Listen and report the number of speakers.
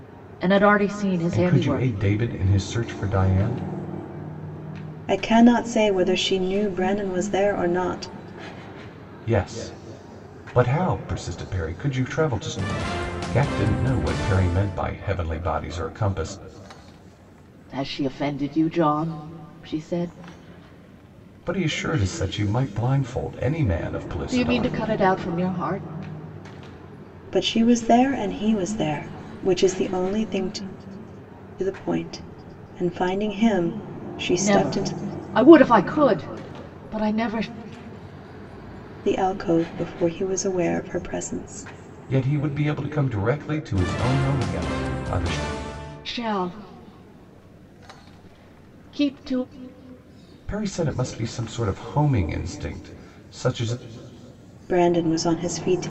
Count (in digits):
3